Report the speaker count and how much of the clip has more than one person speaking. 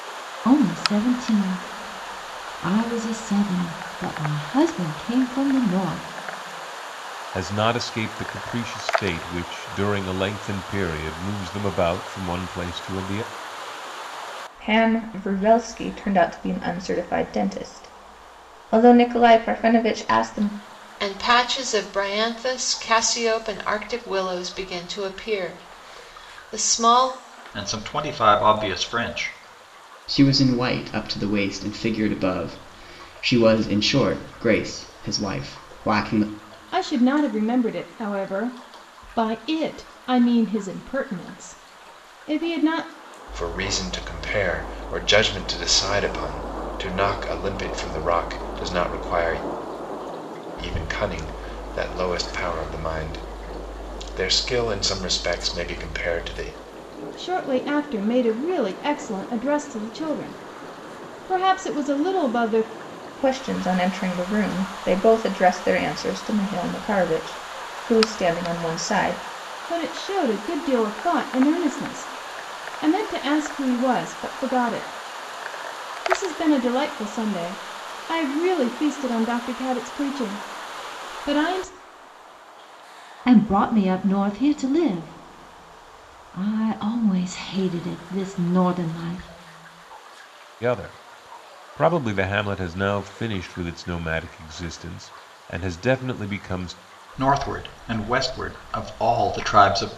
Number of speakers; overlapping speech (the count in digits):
8, no overlap